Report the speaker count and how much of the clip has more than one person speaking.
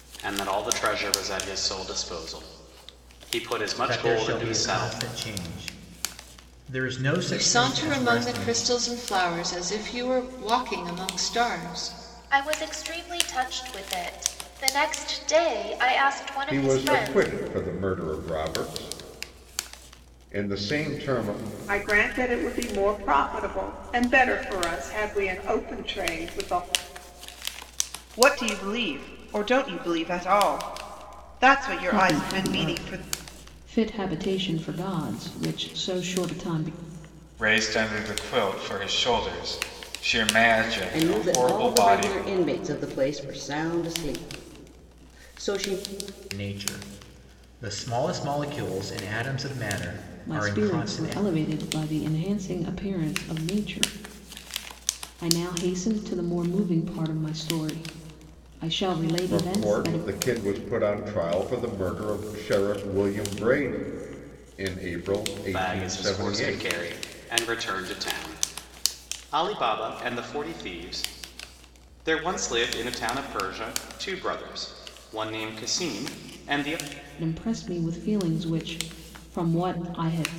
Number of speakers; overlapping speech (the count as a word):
ten, about 11%